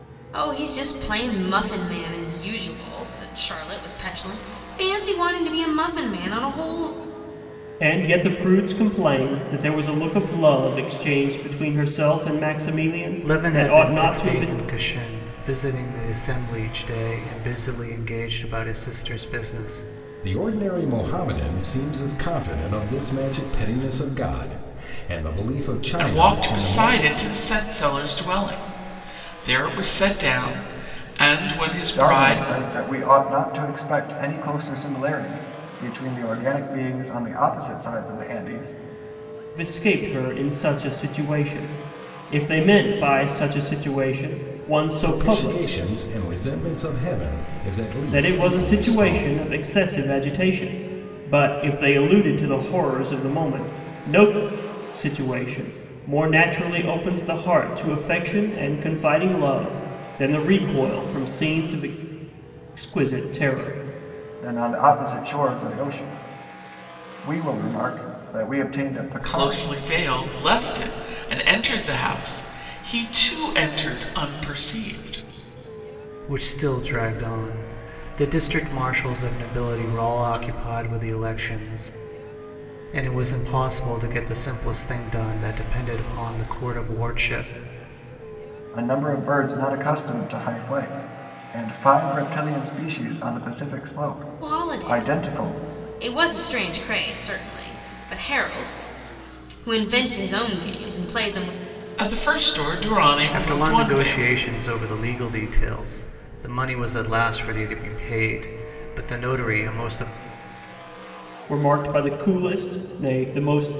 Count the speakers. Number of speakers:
six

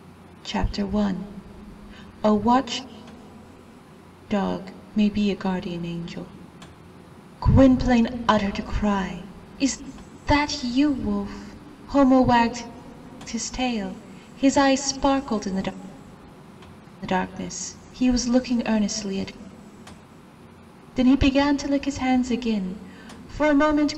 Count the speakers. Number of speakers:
one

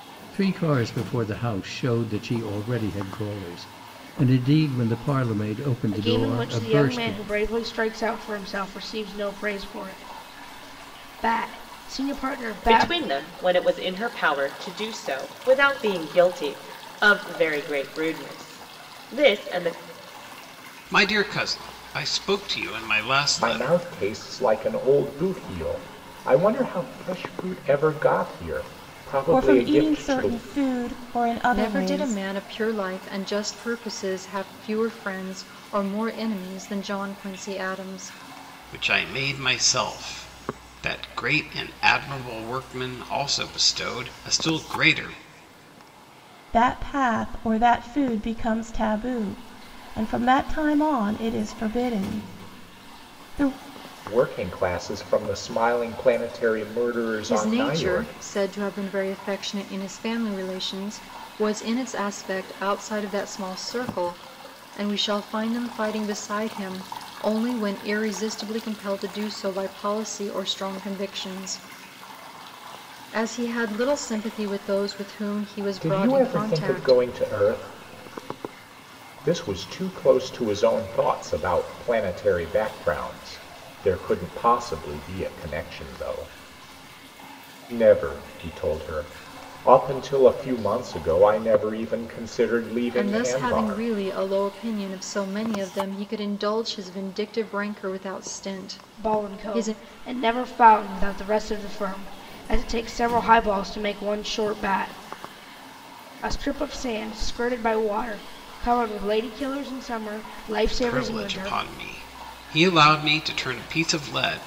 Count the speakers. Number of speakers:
seven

